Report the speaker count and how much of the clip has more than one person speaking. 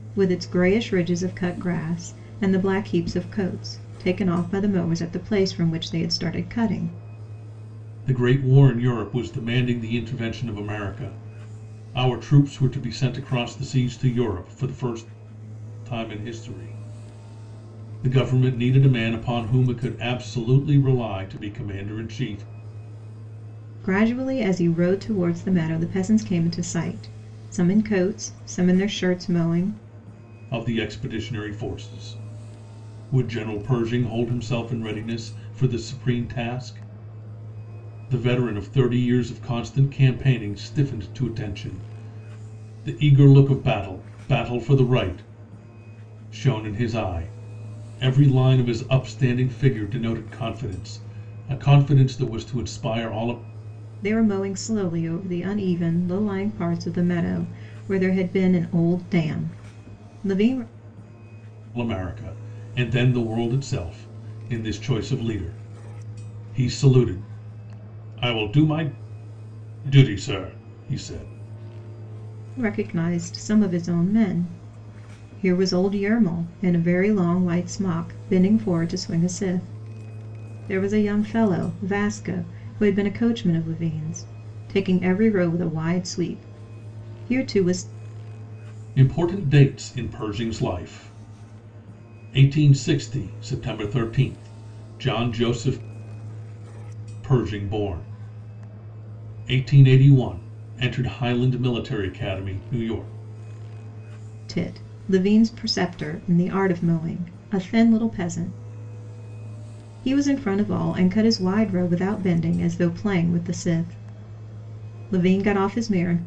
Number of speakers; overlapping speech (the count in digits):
2, no overlap